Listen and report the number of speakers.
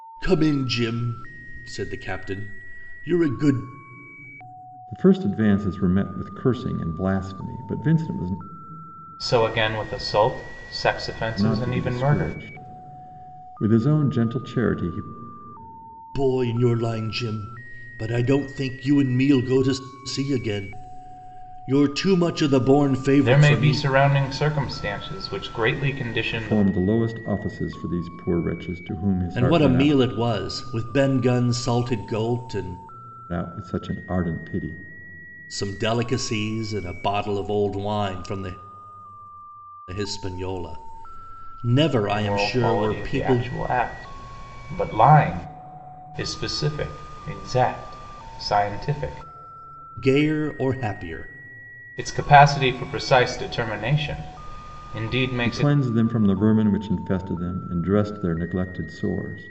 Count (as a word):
three